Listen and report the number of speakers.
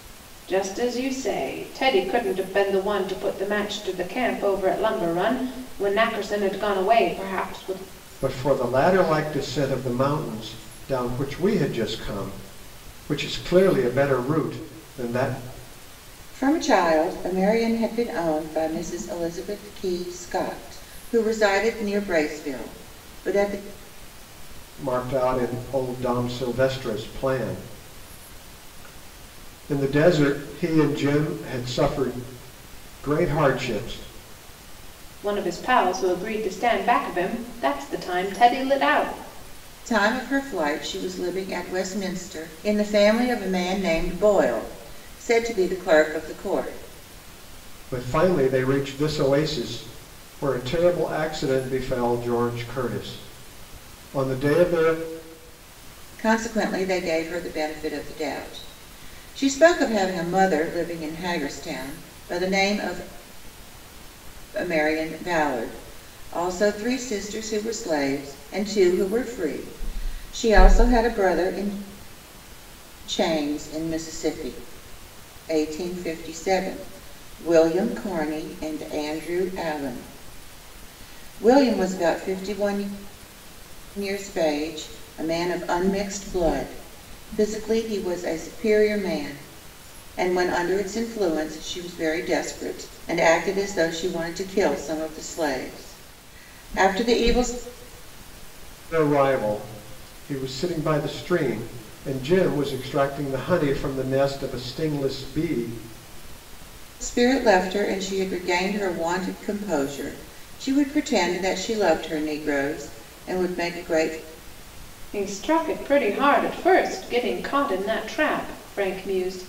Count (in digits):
3